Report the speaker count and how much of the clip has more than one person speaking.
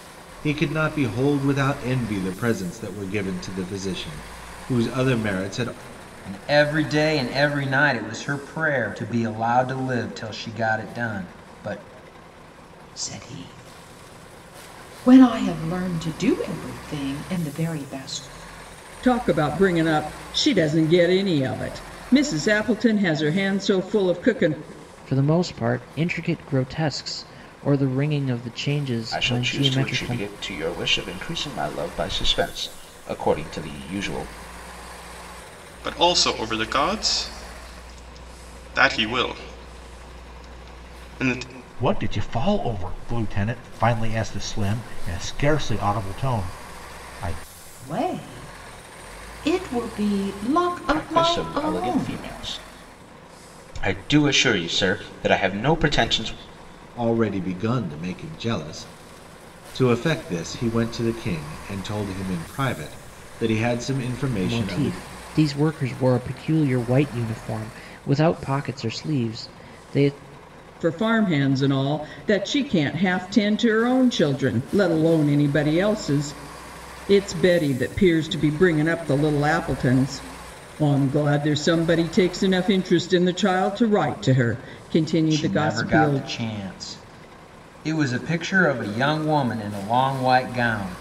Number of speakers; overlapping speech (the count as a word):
eight, about 5%